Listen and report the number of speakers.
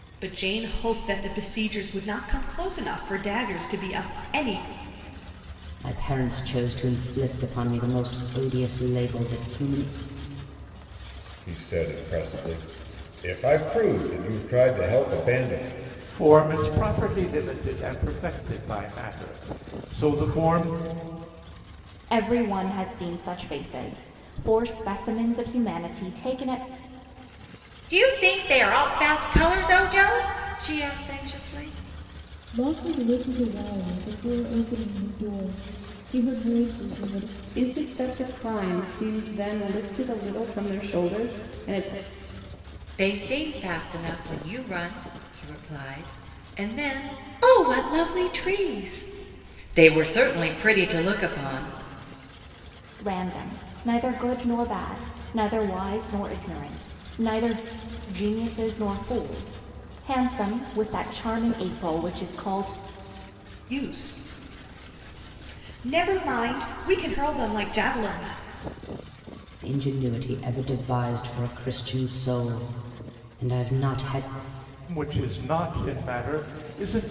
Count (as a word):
eight